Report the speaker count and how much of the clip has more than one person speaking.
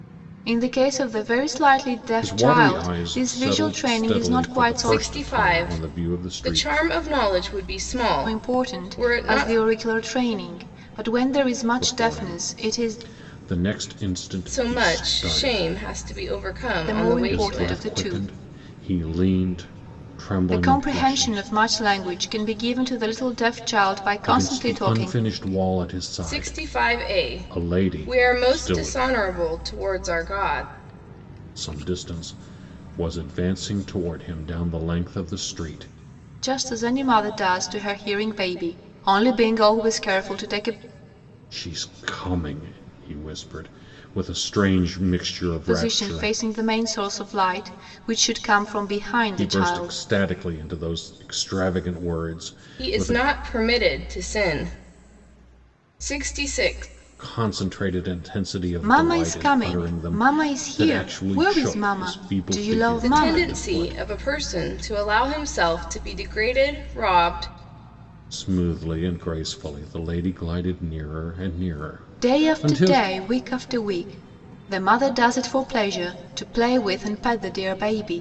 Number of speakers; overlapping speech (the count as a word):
three, about 29%